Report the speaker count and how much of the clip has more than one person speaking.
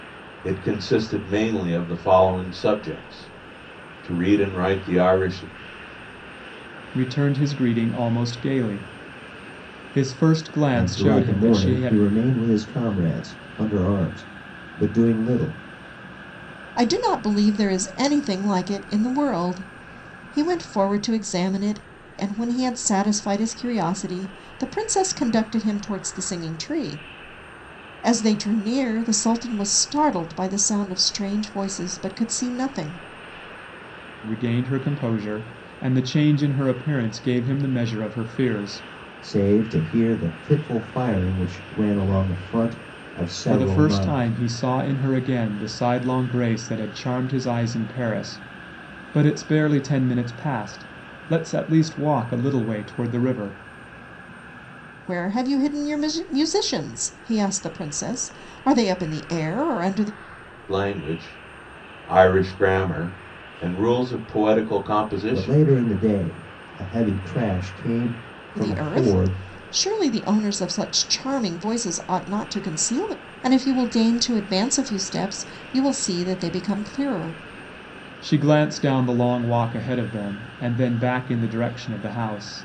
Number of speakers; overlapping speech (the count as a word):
four, about 4%